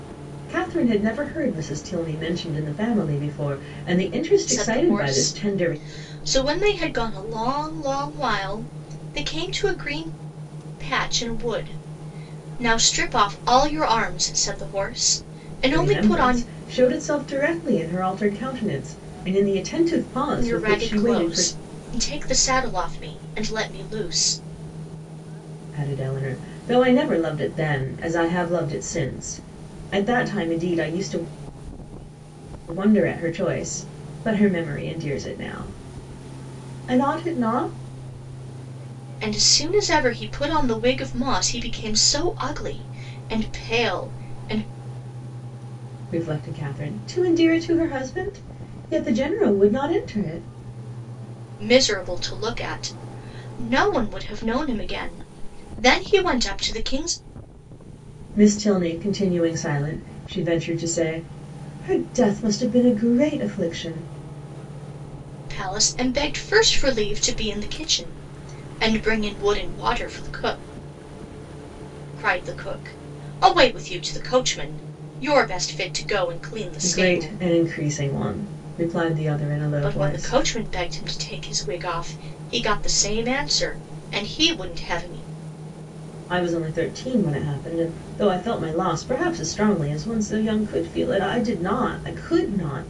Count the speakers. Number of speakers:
2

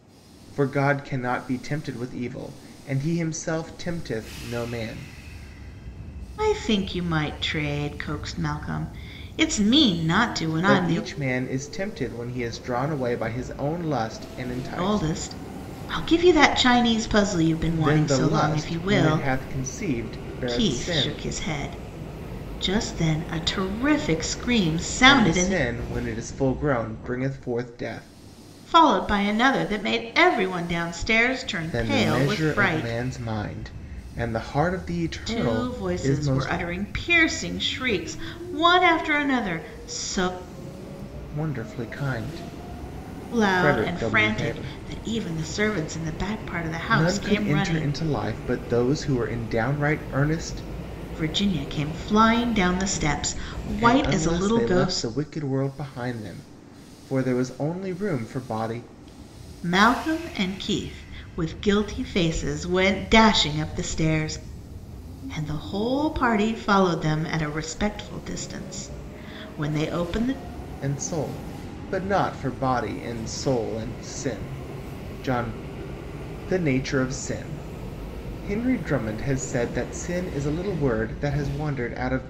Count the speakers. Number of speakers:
2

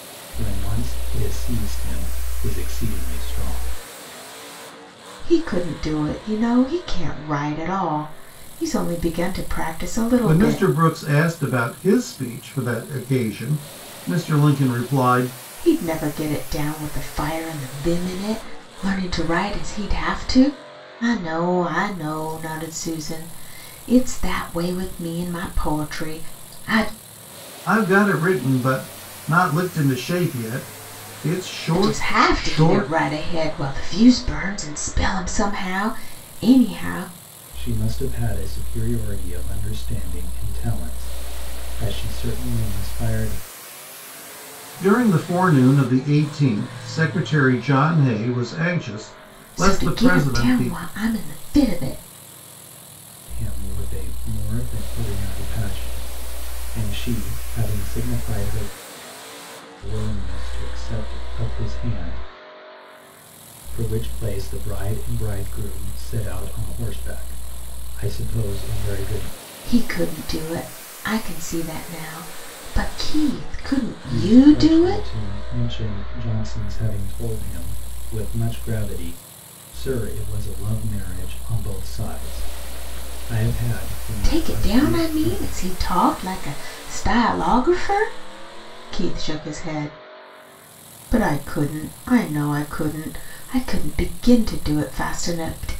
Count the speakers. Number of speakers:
3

